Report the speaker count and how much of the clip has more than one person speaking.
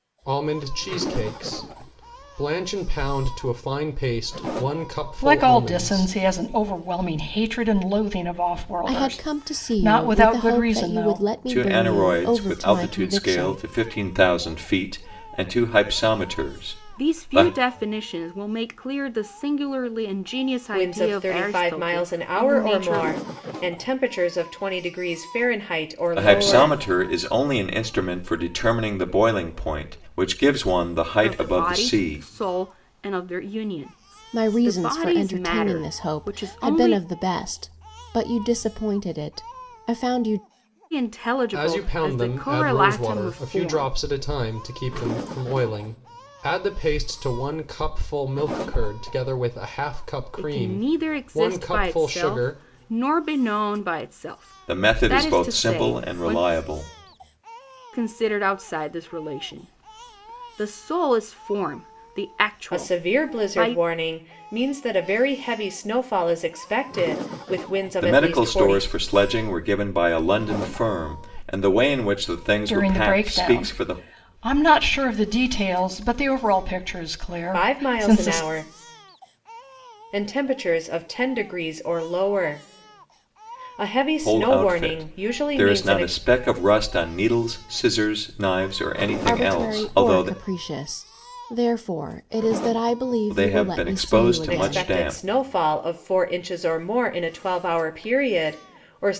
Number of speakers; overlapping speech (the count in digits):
6, about 29%